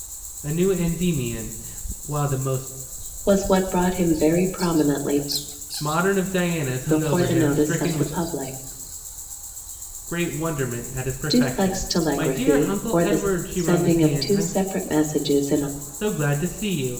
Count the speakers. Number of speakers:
two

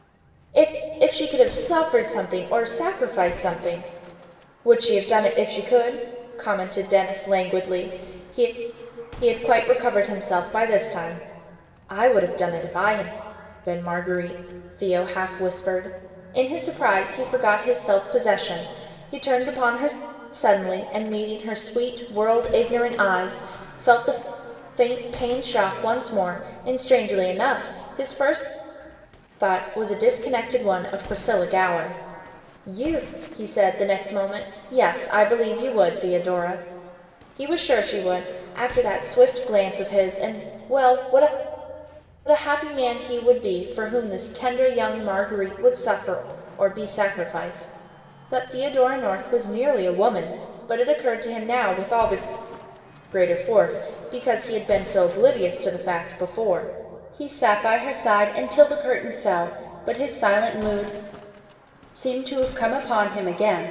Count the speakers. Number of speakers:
one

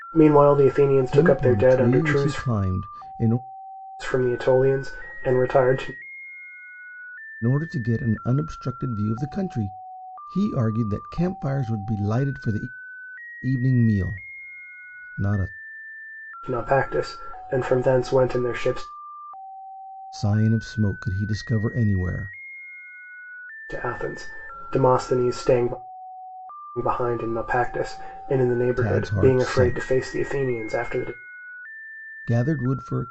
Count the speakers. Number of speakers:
two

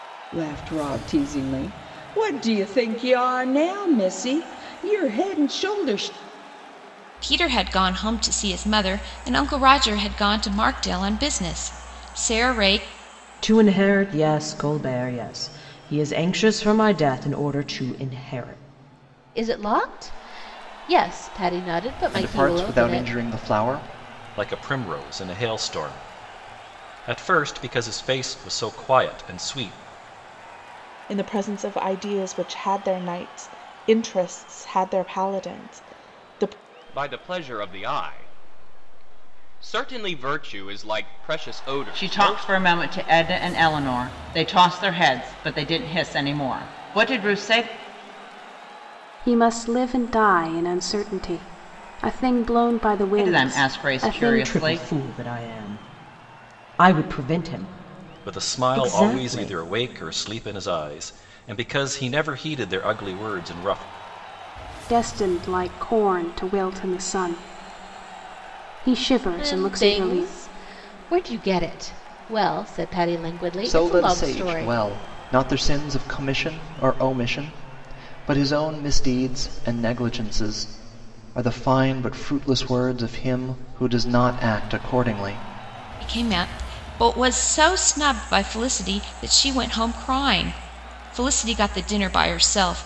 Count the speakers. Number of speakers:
ten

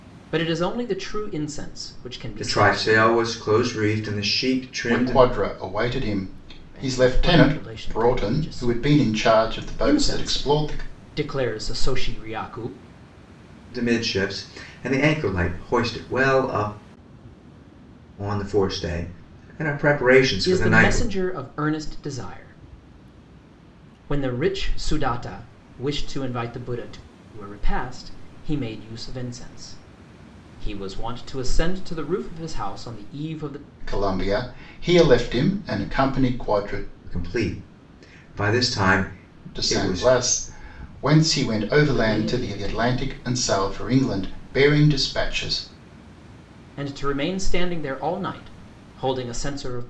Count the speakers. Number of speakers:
three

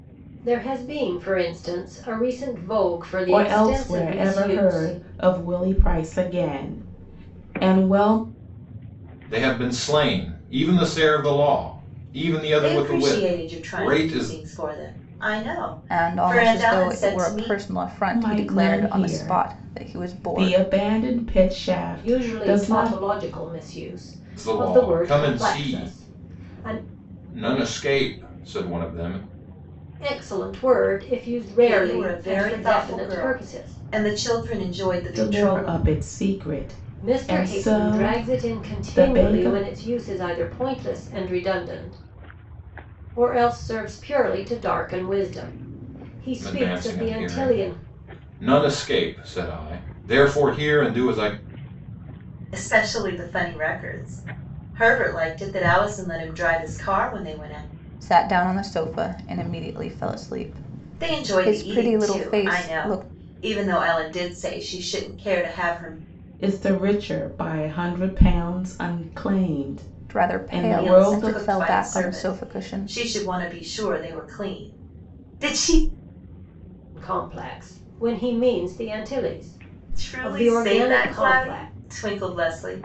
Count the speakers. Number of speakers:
five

